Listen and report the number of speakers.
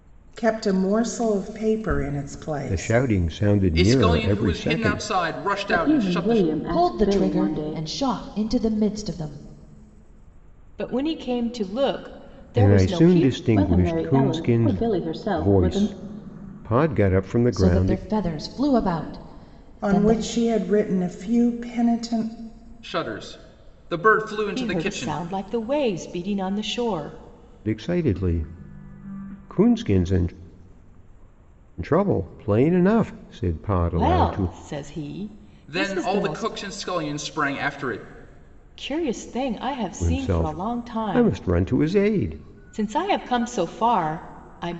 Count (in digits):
6